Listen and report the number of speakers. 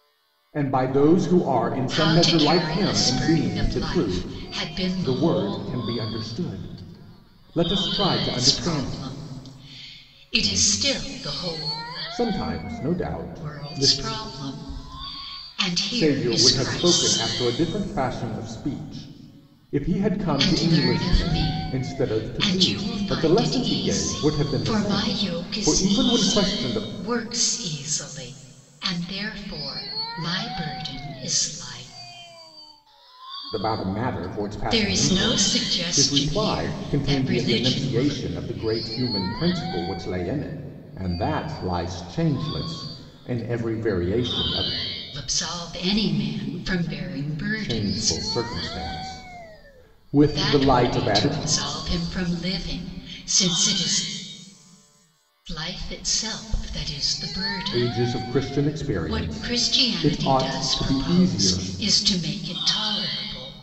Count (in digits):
2